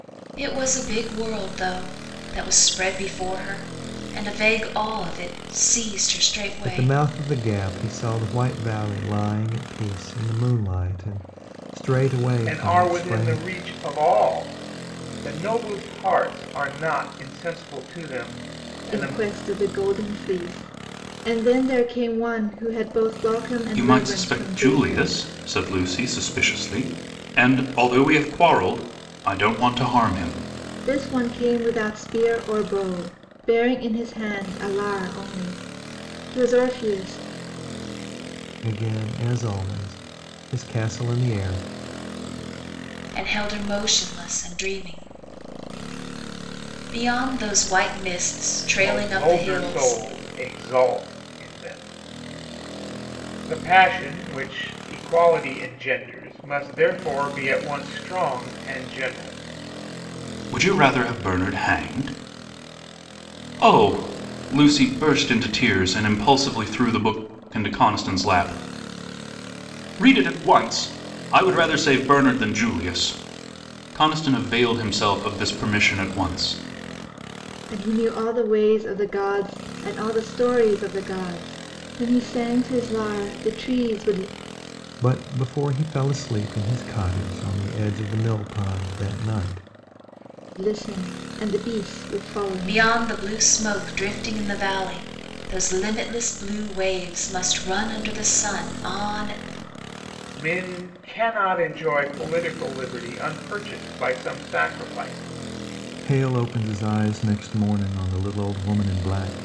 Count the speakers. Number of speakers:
five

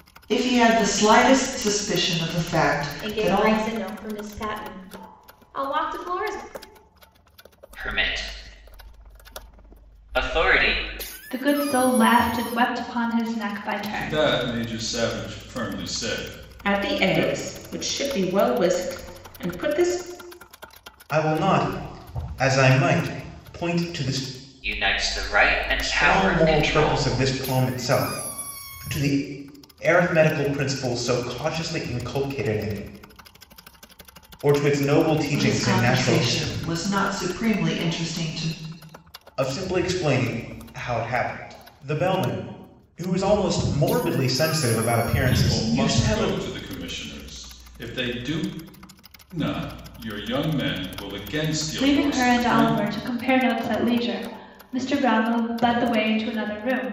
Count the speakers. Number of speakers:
seven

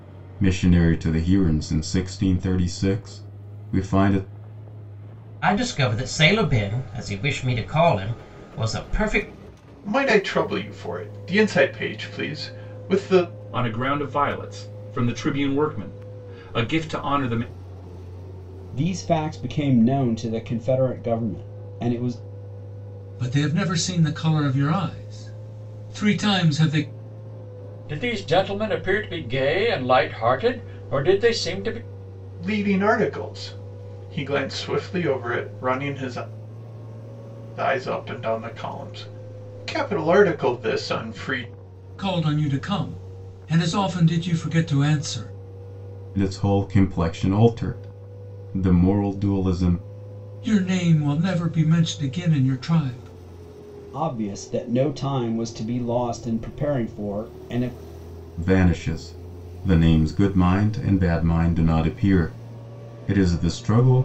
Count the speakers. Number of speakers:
seven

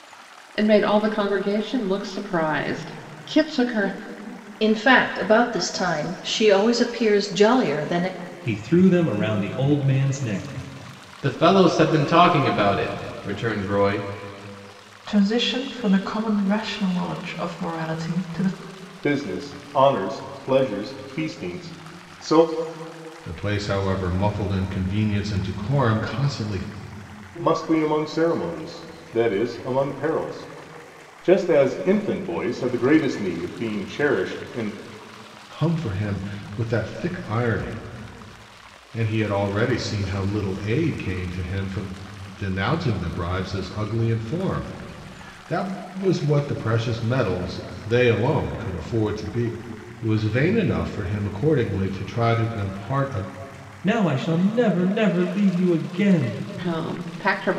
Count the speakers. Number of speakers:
seven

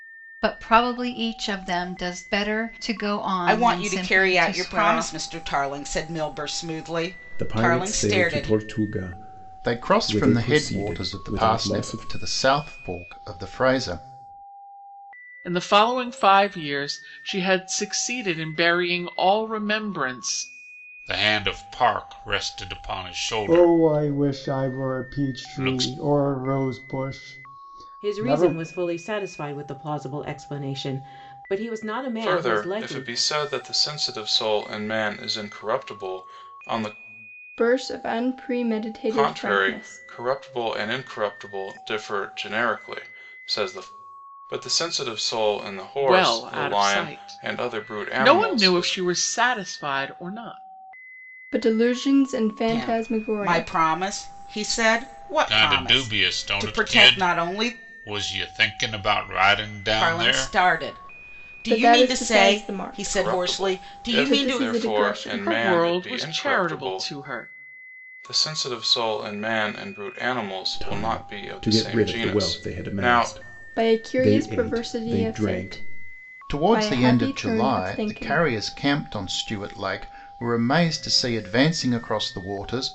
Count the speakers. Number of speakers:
ten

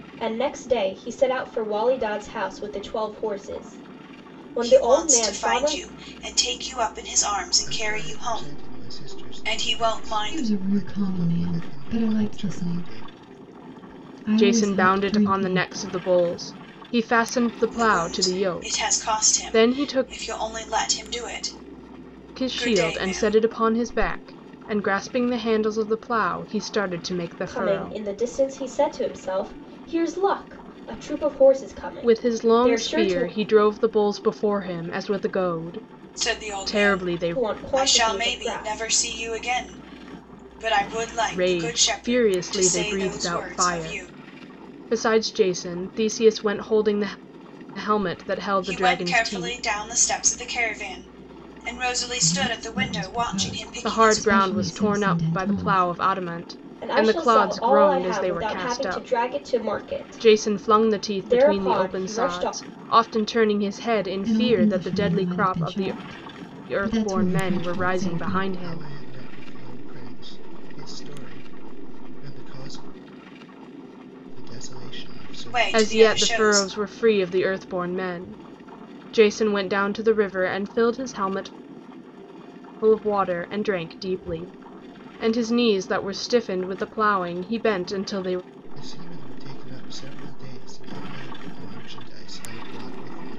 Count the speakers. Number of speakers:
five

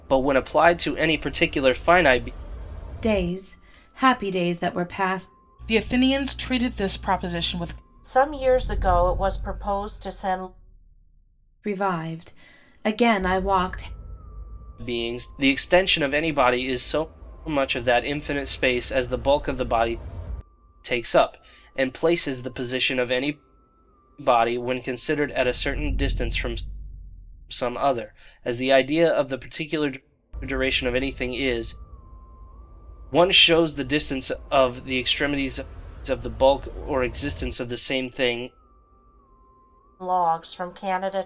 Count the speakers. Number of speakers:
four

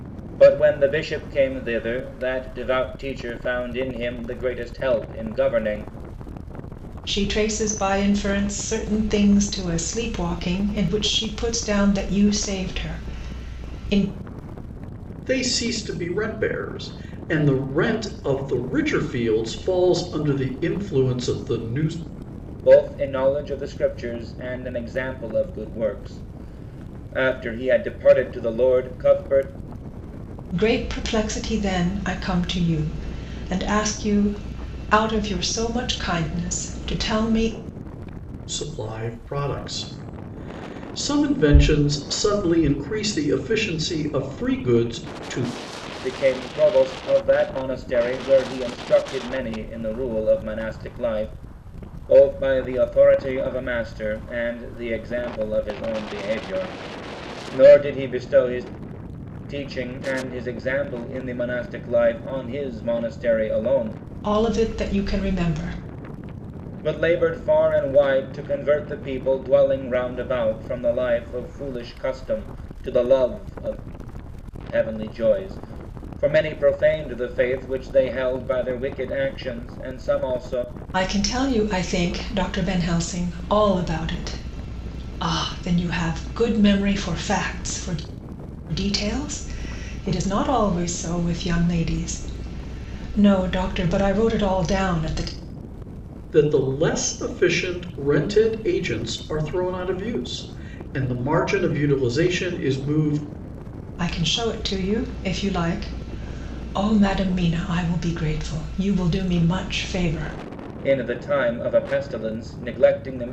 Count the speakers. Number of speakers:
three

